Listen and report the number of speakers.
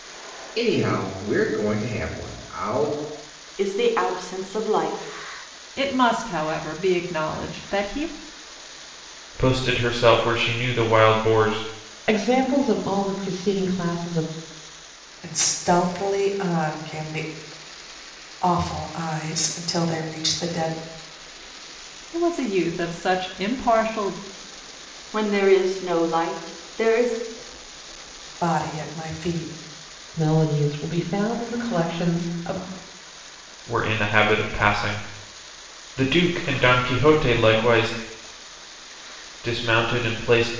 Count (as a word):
six